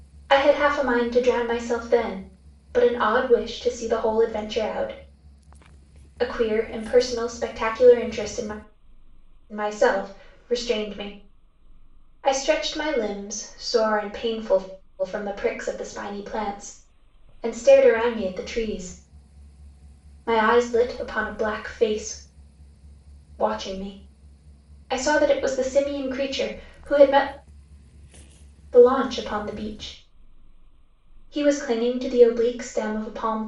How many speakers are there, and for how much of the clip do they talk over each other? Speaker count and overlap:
one, no overlap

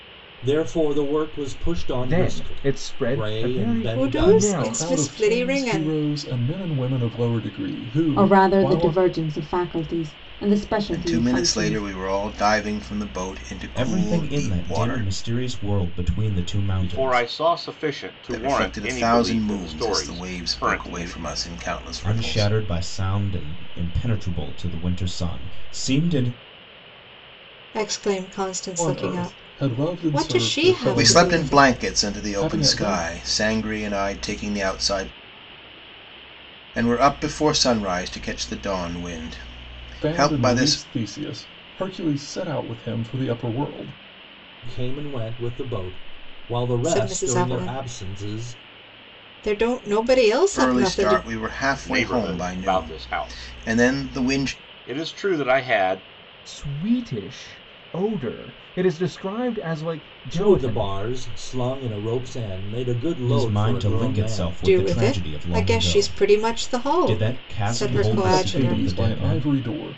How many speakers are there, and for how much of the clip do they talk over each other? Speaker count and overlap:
eight, about 41%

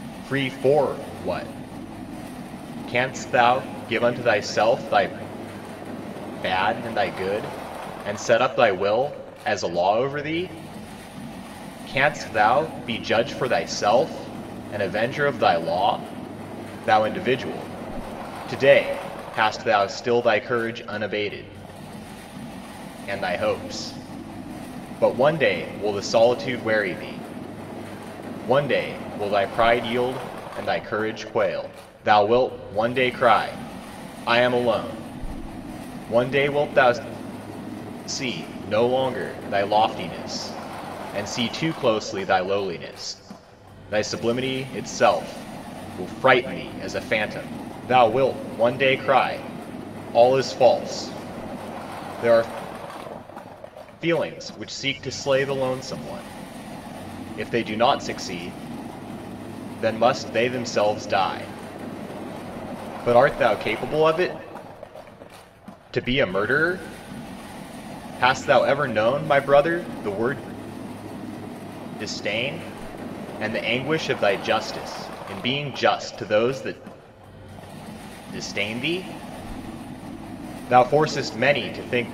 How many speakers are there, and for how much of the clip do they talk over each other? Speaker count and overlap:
one, no overlap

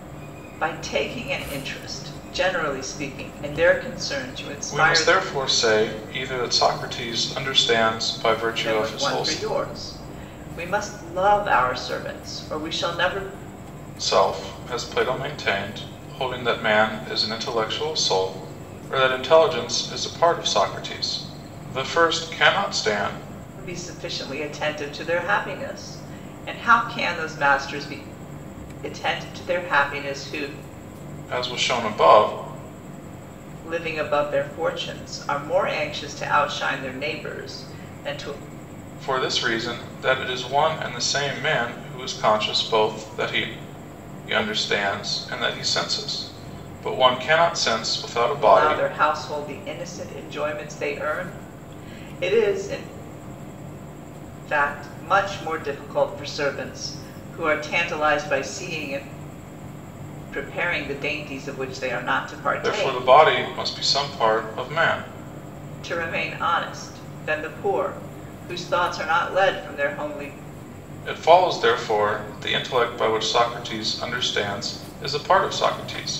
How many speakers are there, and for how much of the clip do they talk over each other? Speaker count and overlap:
two, about 3%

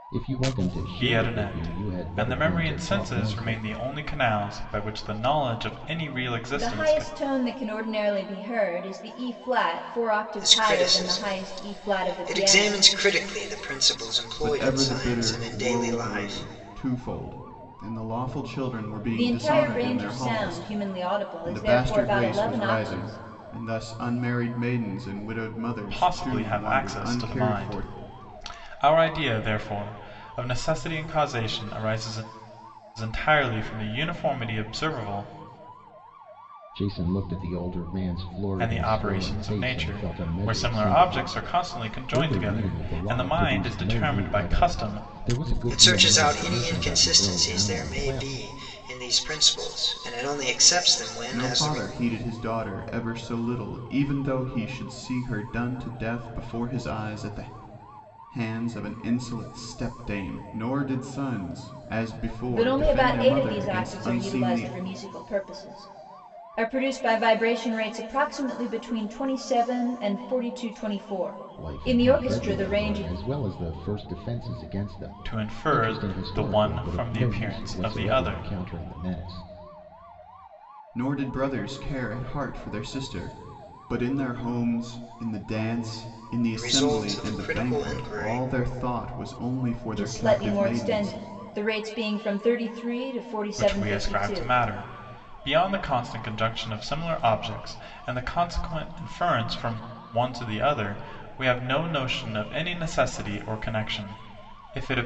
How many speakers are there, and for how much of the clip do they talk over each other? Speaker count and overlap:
five, about 32%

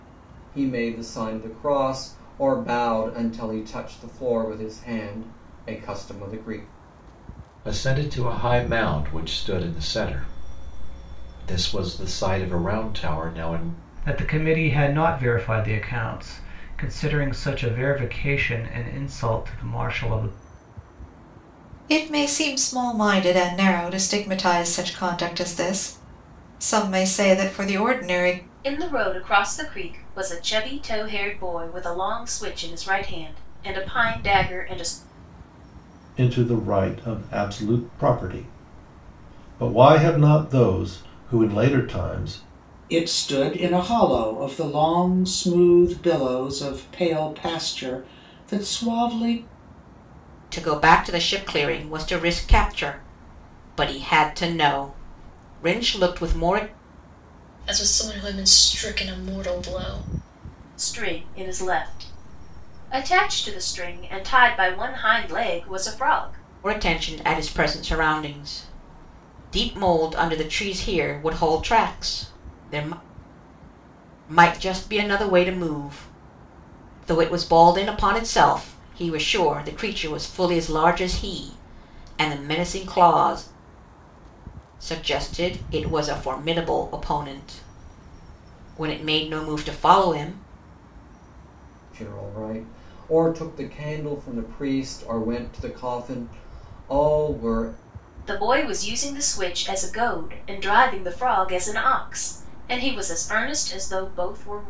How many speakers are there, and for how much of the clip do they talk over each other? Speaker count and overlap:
nine, no overlap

